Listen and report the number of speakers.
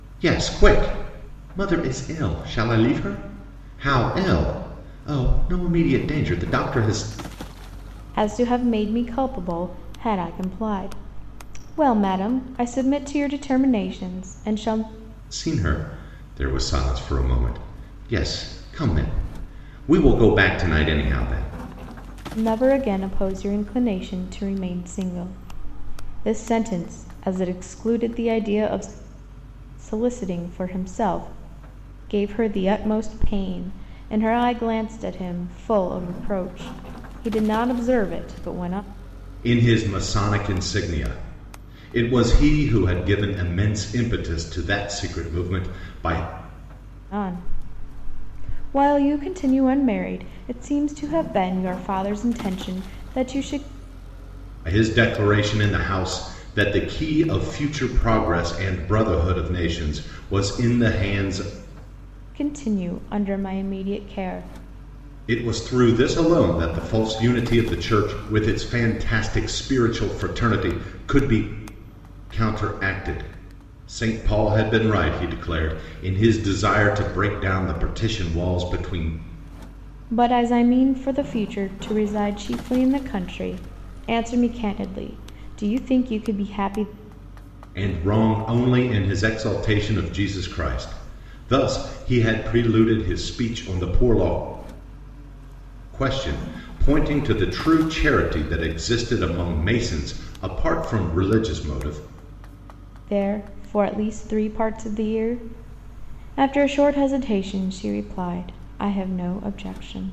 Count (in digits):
2